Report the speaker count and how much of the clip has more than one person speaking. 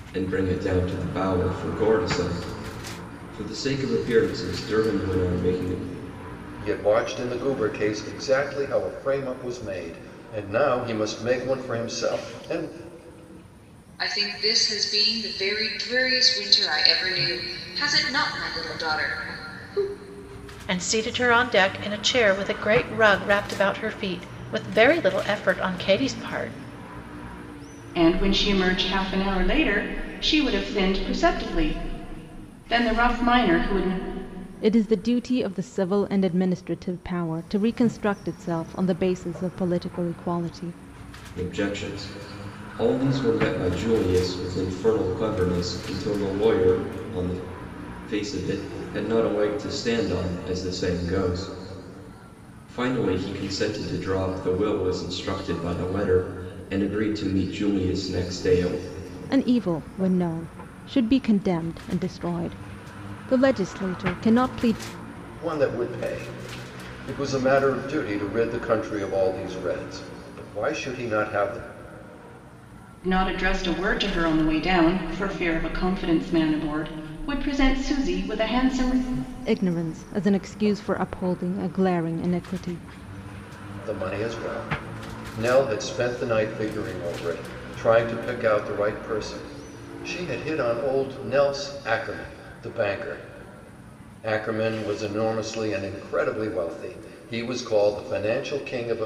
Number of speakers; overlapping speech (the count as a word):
six, no overlap